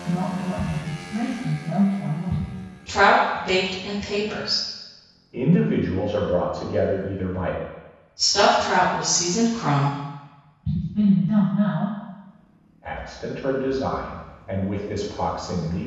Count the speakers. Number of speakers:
three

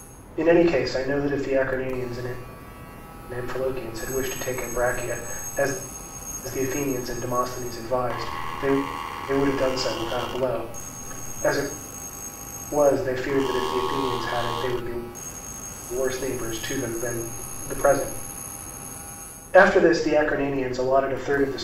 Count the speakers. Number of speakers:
one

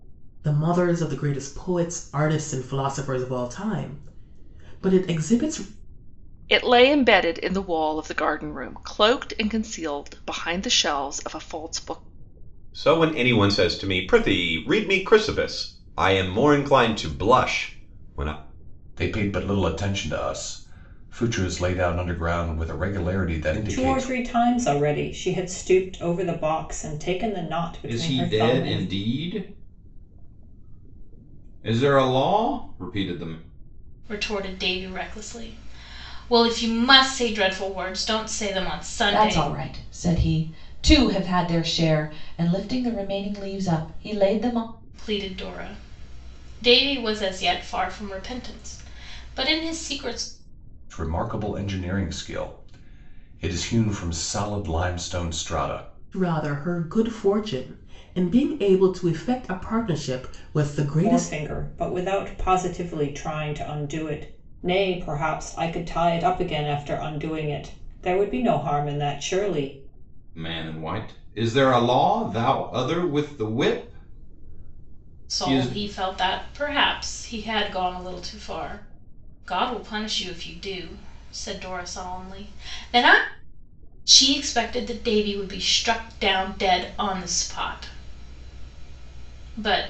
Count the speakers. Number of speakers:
eight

